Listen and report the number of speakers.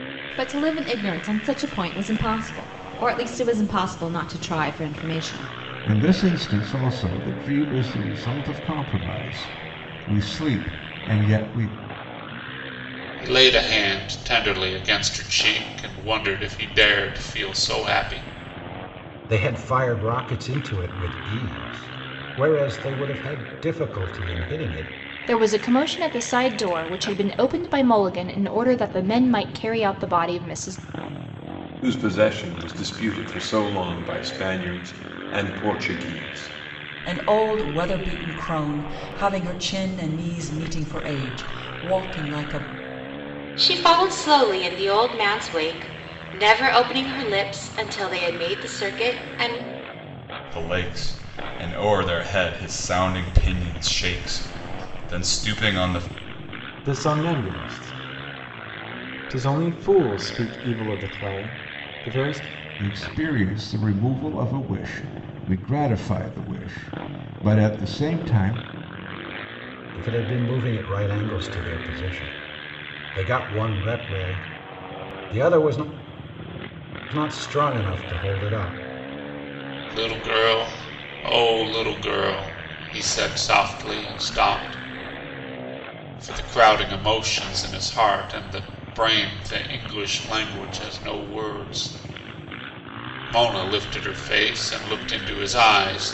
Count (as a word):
ten